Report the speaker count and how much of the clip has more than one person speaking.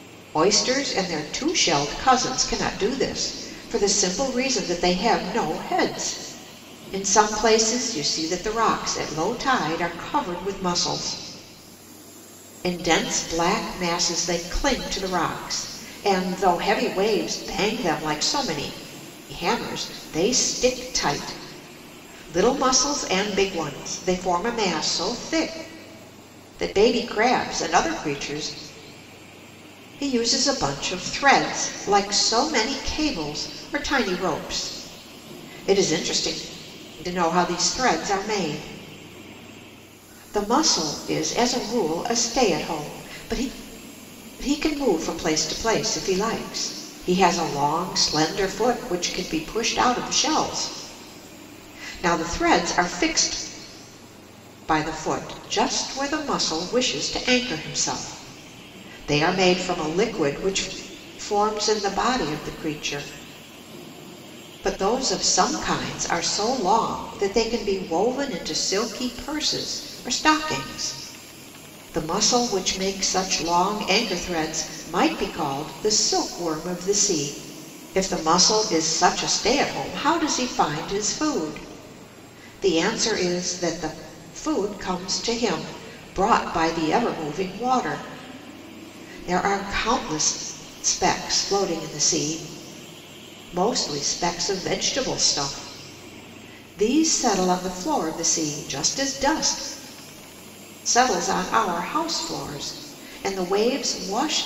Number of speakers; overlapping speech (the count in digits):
1, no overlap